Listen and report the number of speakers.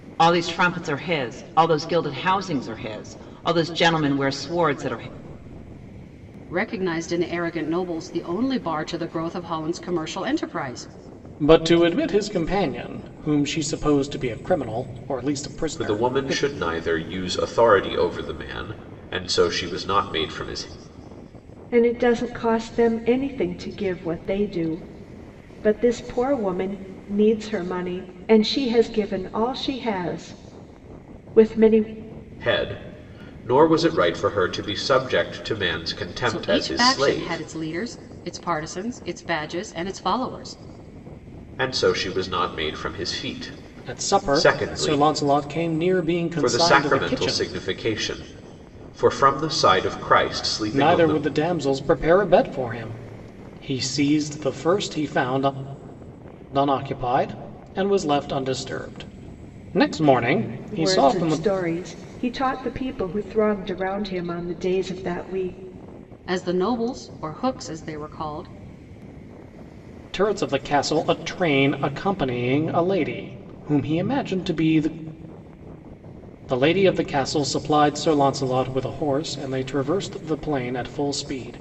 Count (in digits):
5